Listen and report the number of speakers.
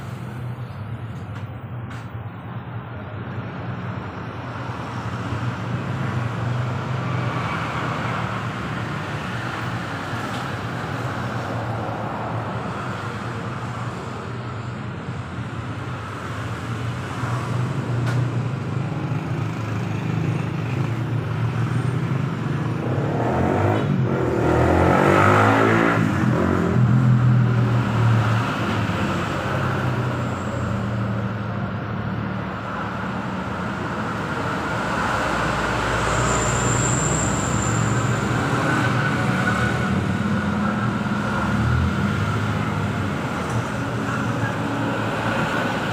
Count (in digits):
0